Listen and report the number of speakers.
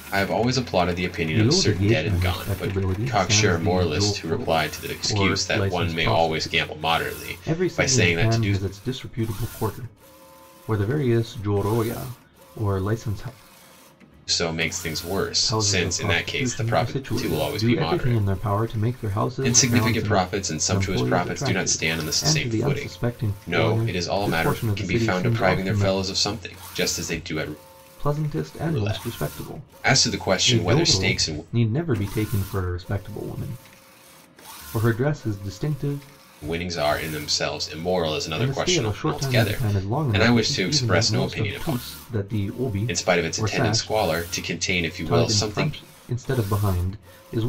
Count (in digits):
2